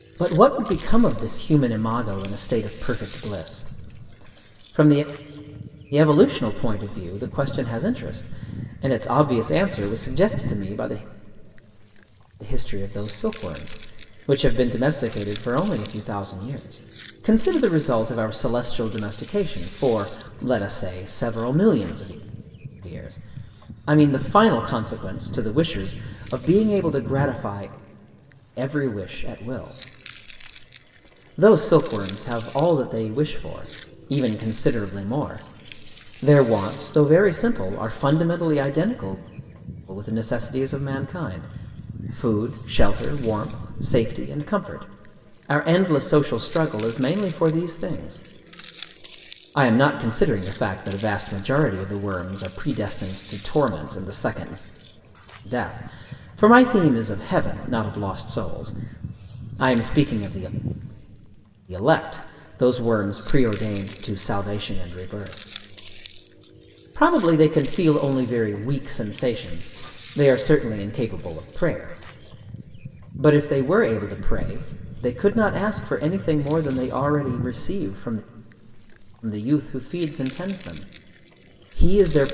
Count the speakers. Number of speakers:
1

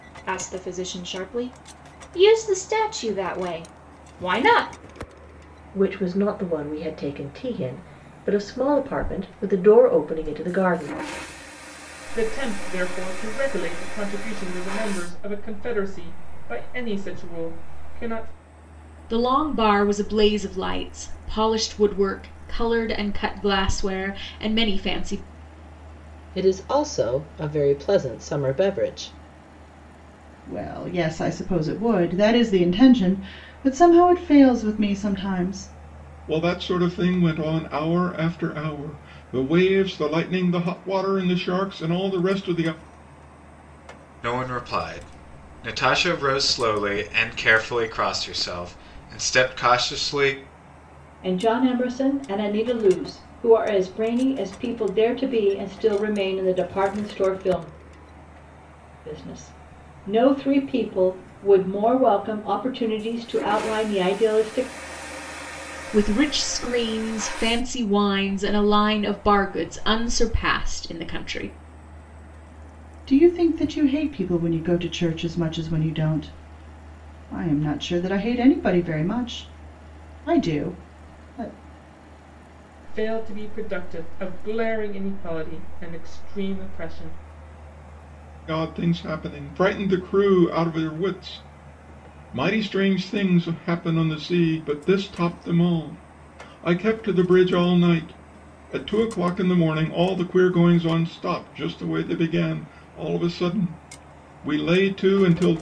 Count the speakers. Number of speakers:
9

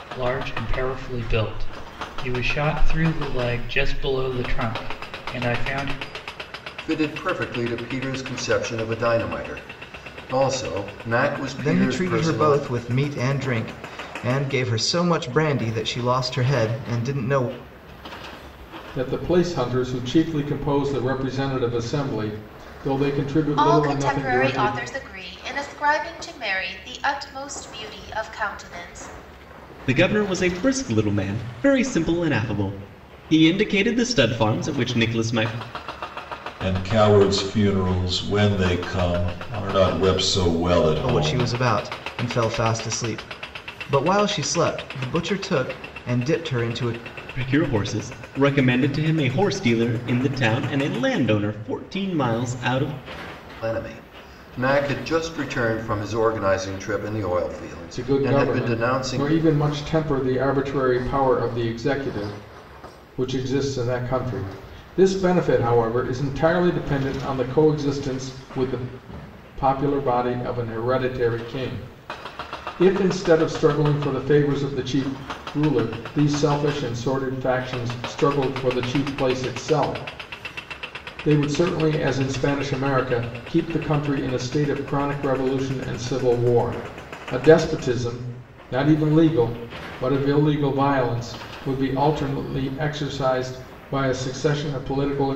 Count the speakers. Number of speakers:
7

